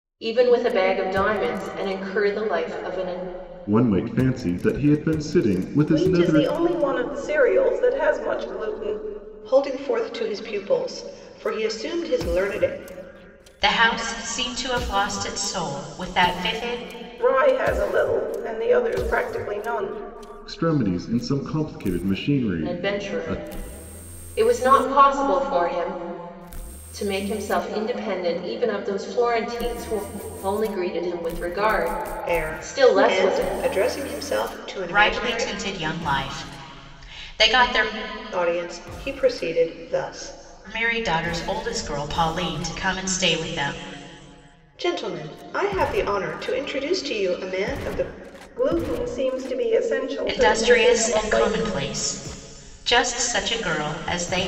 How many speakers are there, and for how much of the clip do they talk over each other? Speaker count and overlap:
5, about 9%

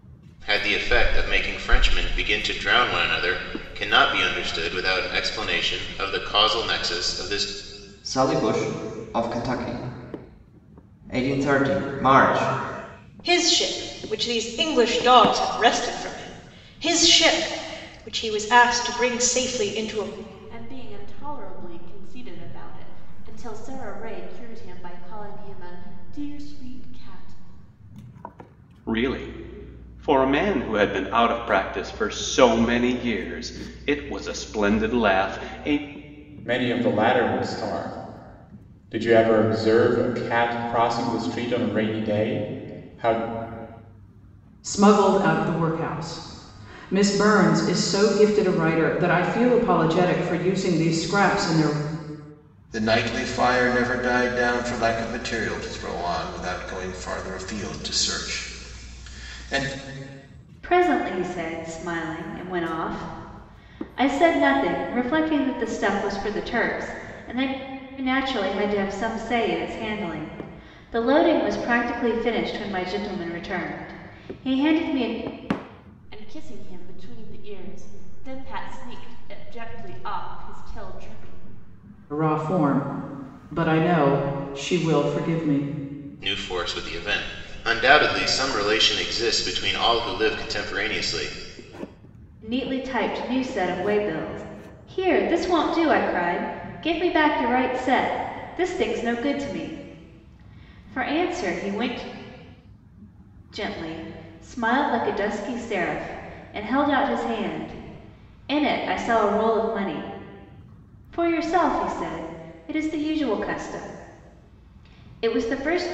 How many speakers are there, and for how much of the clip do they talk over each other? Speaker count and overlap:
9, no overlap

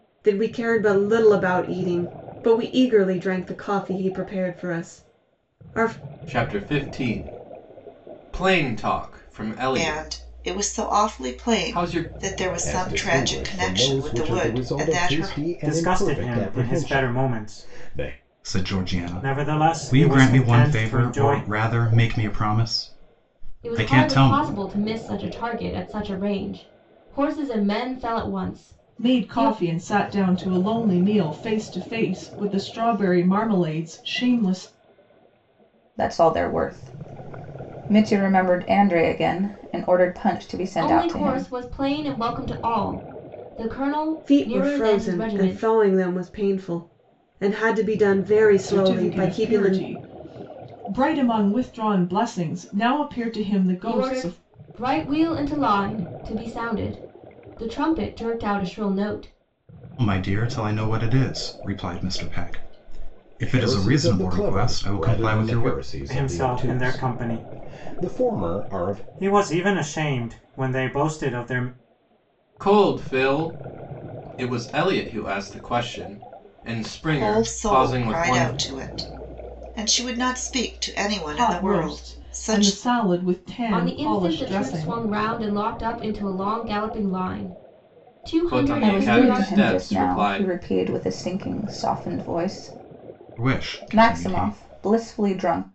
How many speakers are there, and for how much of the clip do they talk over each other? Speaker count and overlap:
9, about 30%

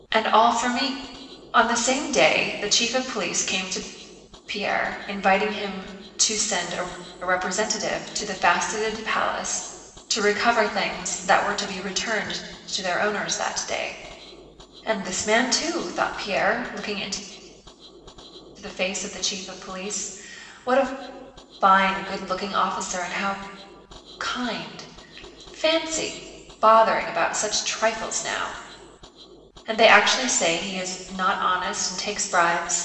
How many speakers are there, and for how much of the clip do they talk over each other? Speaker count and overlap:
1, no overlap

